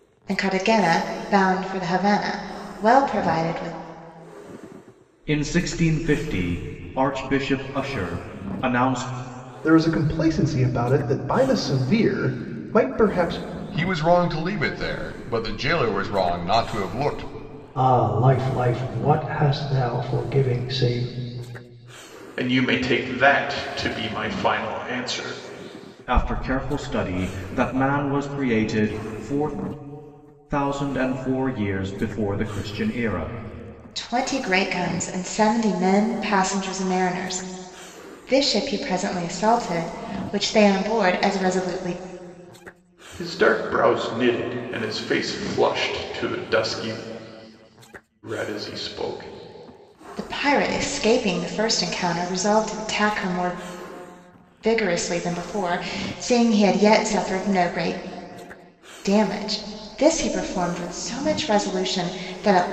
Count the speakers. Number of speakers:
6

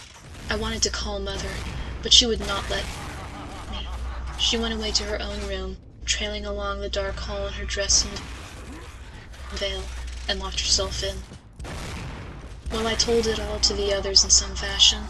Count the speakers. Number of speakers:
1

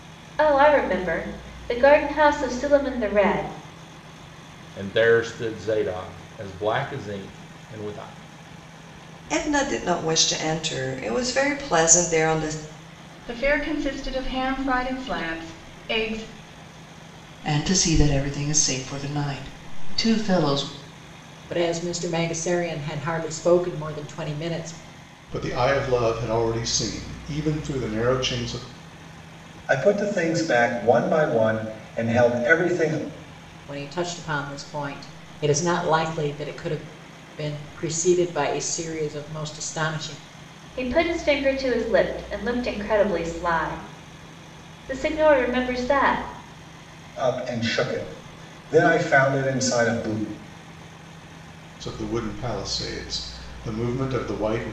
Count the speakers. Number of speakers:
8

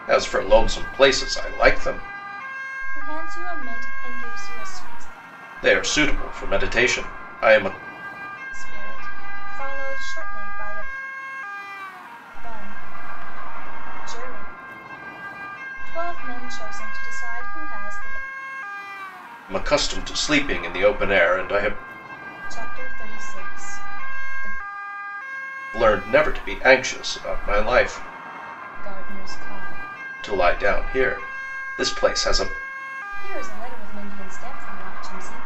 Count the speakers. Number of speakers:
2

